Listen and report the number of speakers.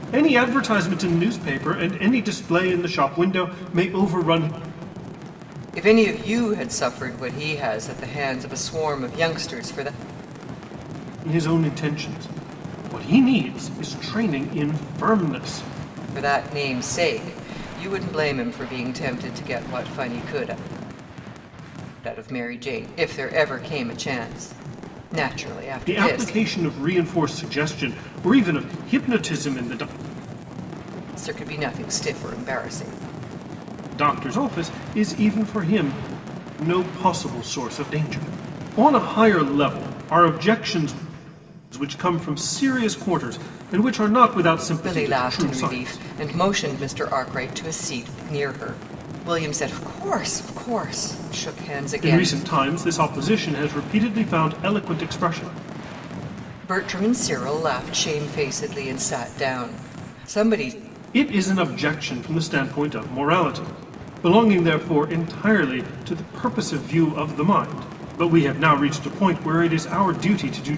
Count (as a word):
two